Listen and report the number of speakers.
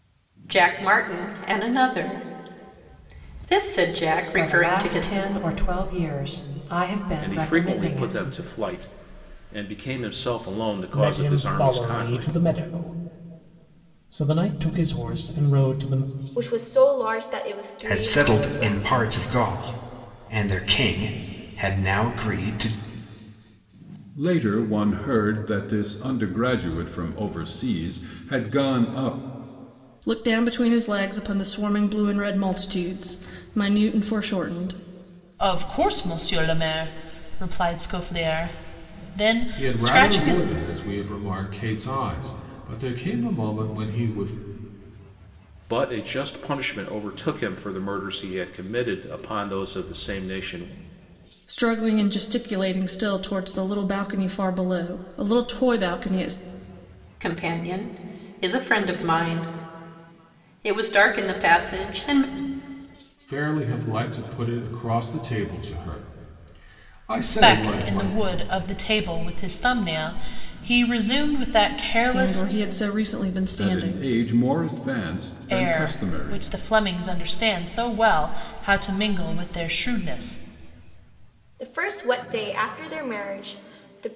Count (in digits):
10